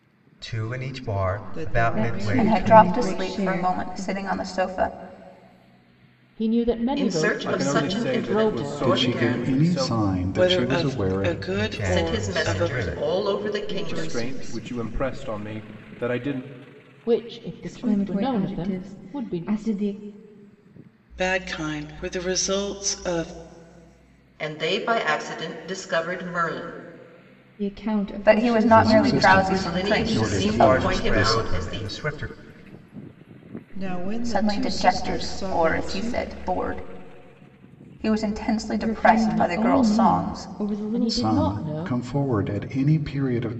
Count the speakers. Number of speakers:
nine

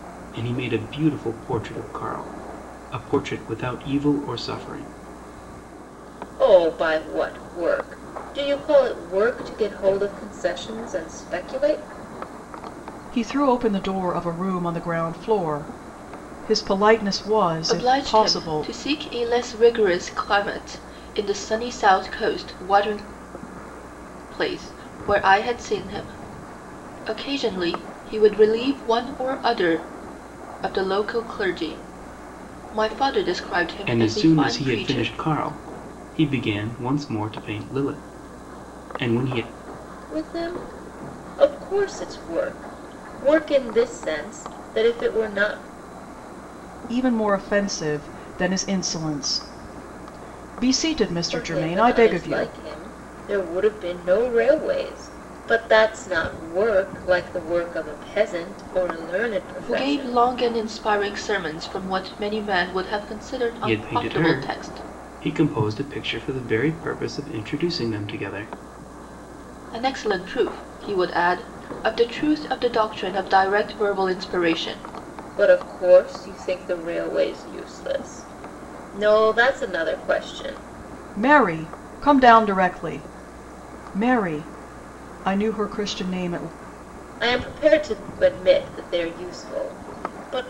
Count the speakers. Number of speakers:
four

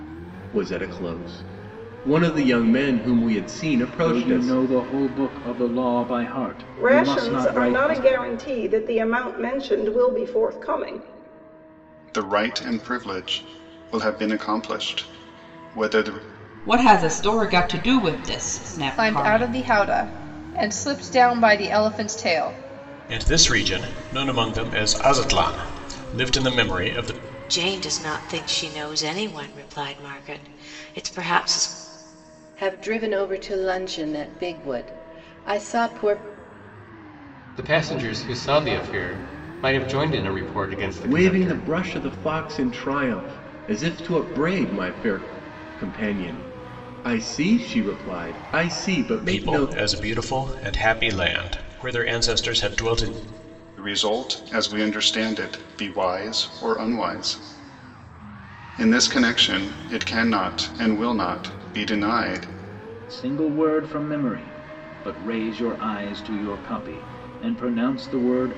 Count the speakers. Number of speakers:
ten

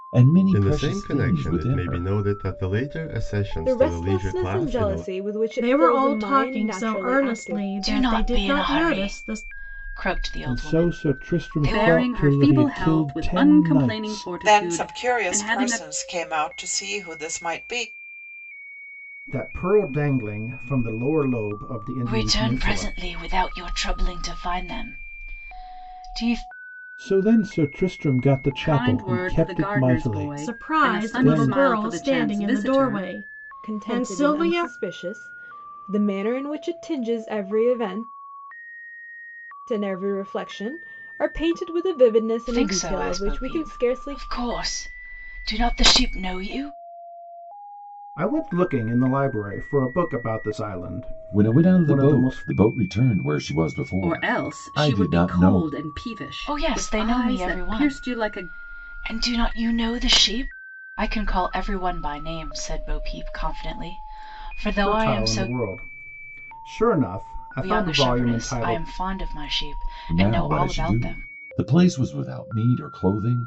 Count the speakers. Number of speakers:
nine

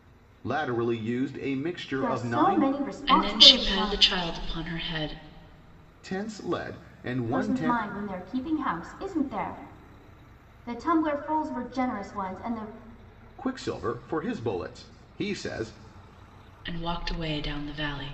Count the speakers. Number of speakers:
three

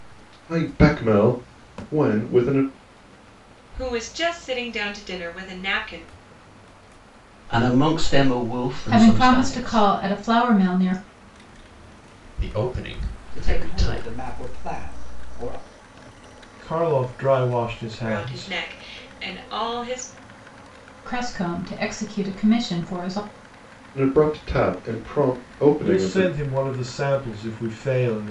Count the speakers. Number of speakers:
seven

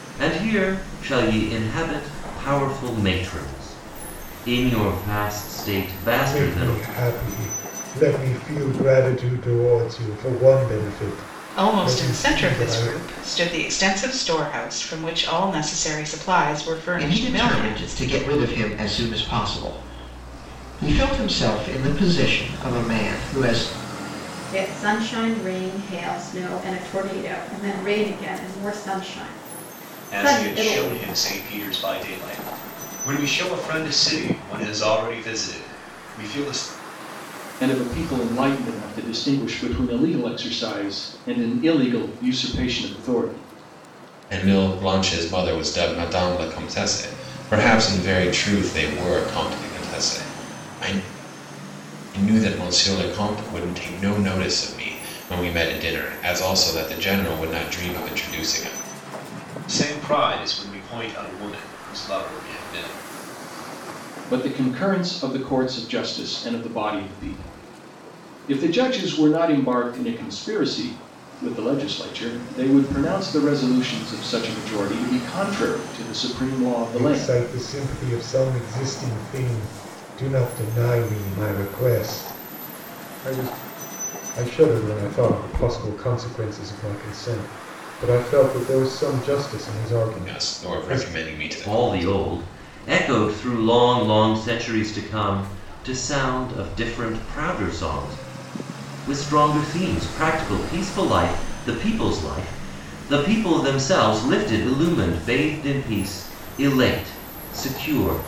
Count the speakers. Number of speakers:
eight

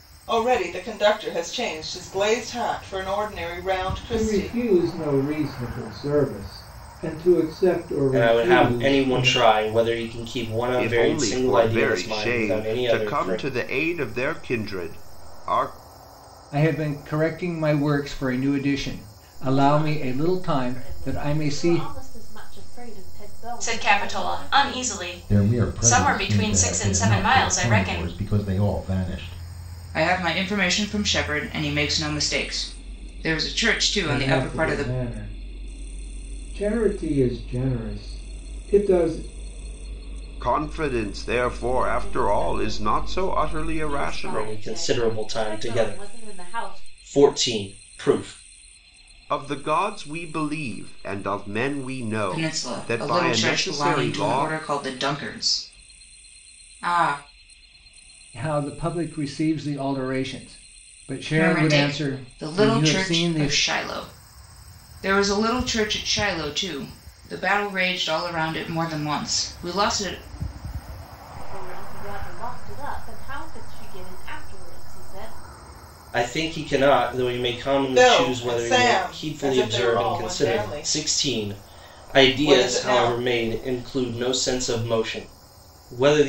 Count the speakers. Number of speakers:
nine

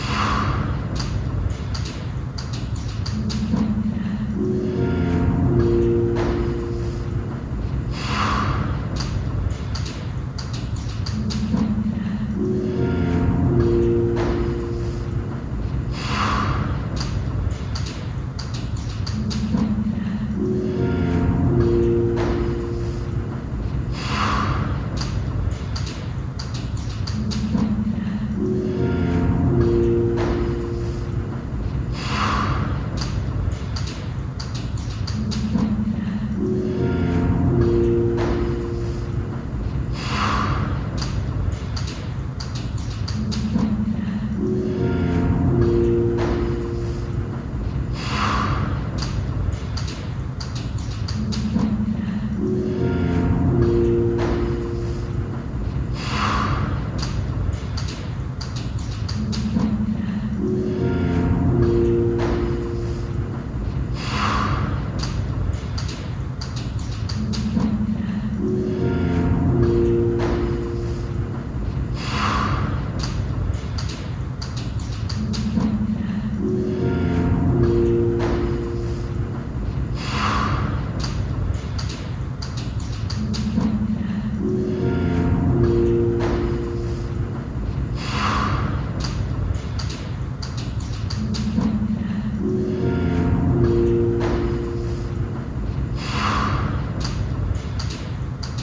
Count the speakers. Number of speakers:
zero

